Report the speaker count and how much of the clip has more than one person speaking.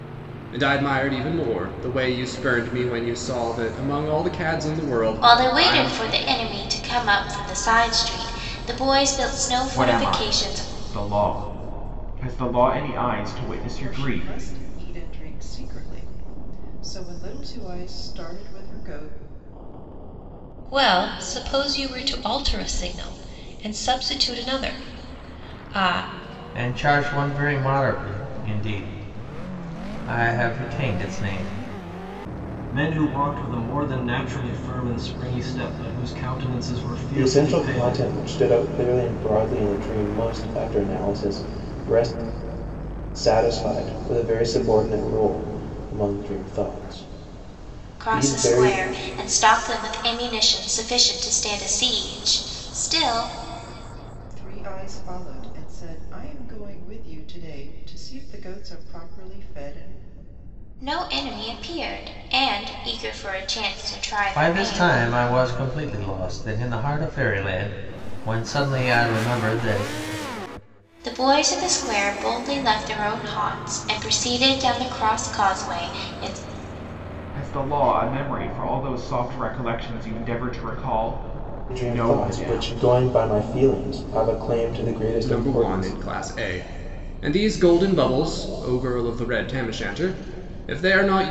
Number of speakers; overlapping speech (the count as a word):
eight, about 8%